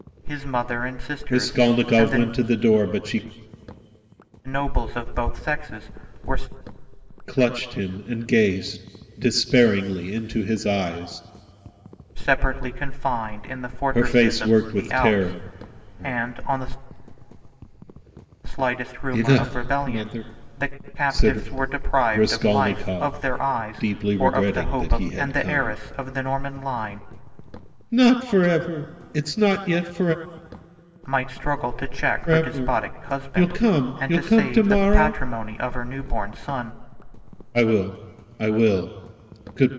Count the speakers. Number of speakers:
2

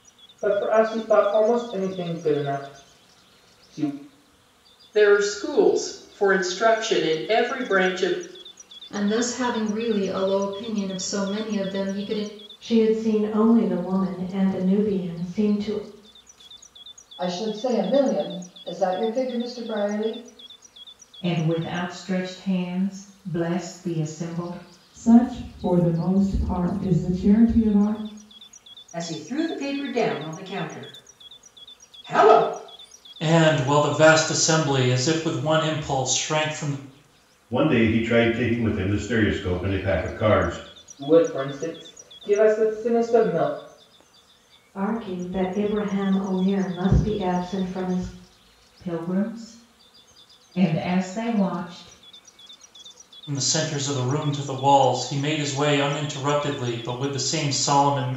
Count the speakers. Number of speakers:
10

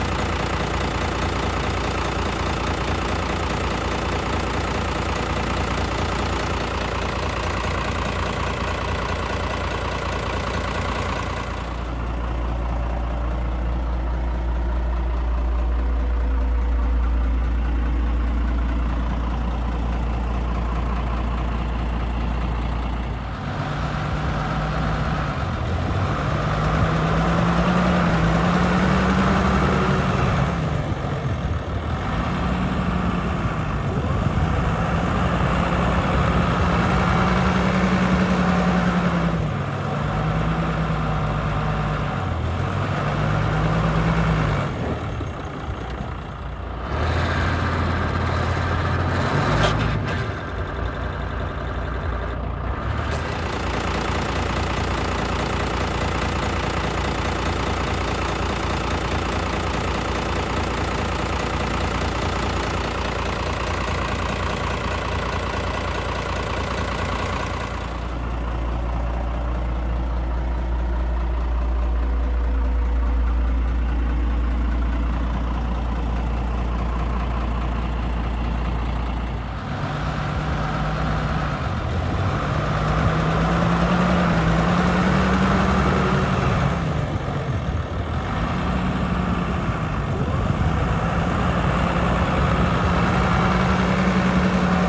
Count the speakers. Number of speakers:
0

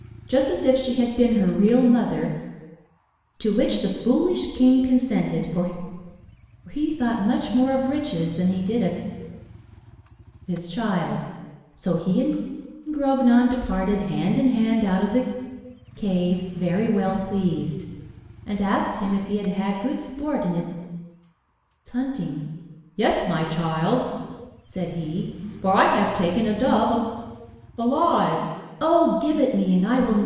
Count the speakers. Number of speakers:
1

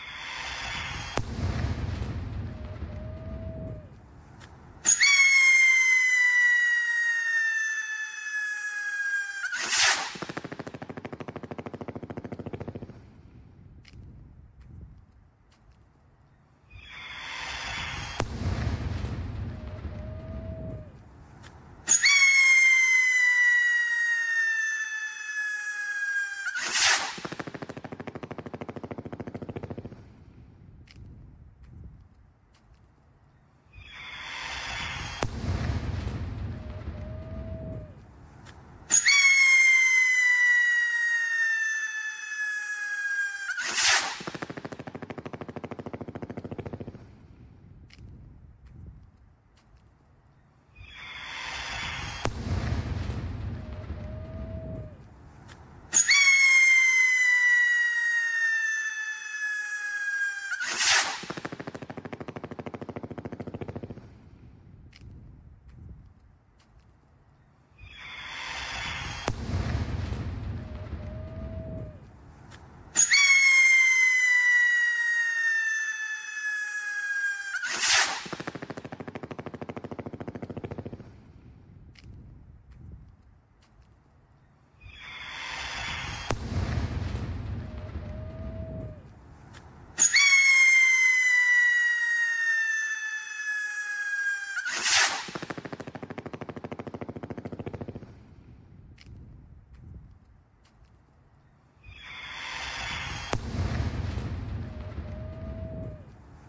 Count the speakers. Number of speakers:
0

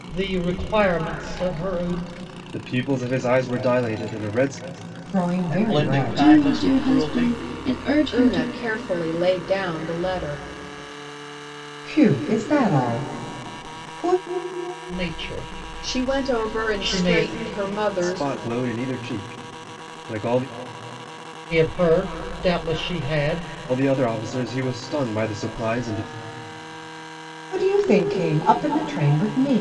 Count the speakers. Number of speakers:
6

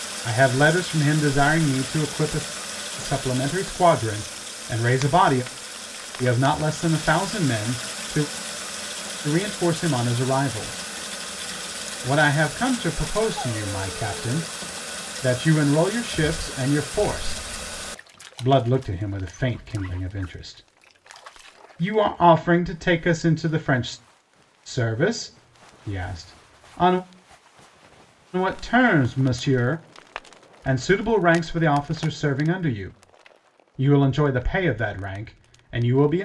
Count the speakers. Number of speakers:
1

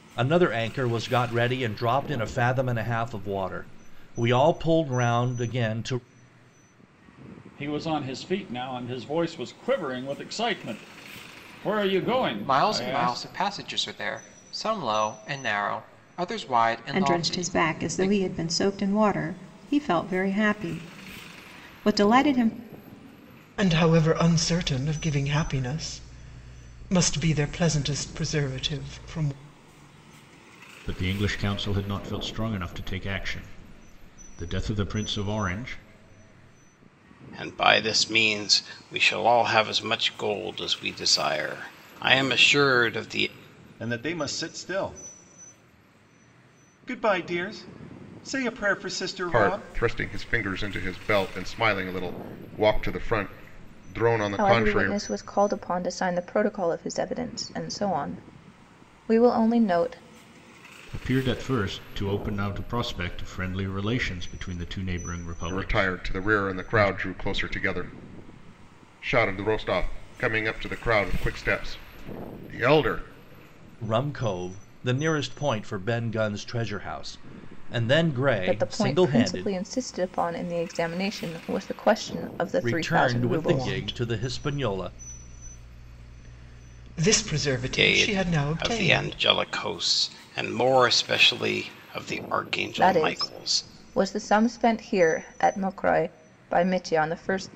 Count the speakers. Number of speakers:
10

